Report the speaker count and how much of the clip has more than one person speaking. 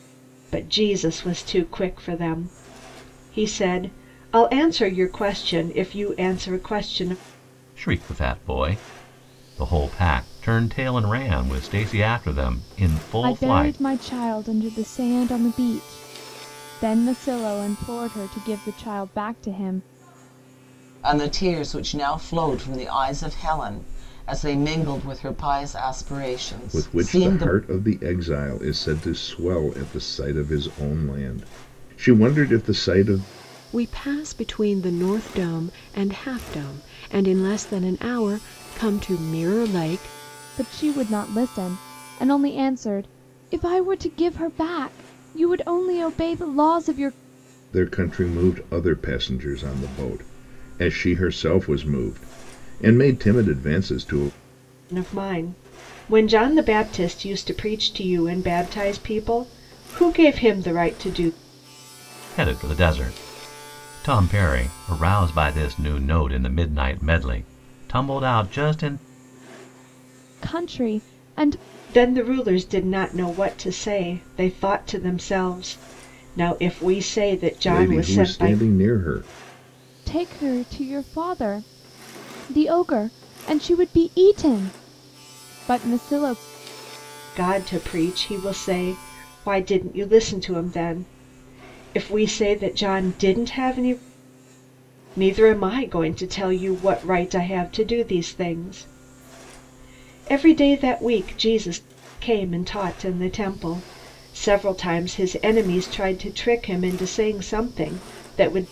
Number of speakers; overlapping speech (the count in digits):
6, about 2%